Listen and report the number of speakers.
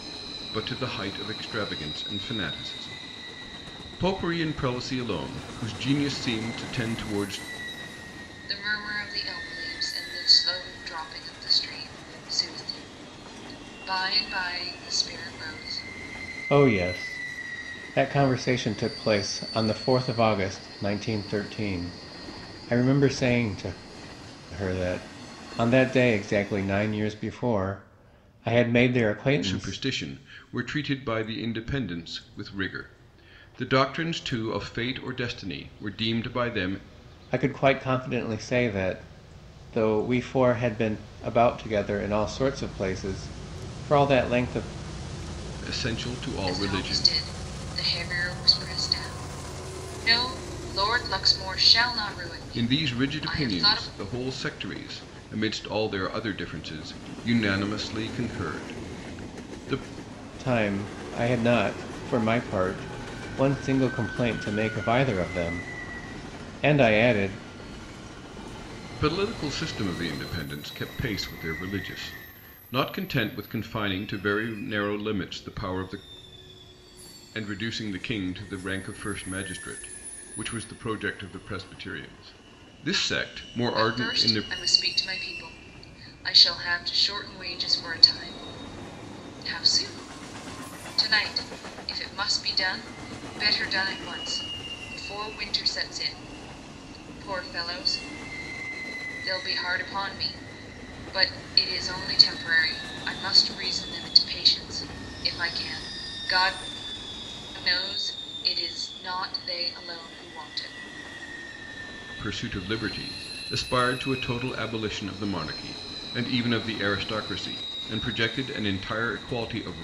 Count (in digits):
3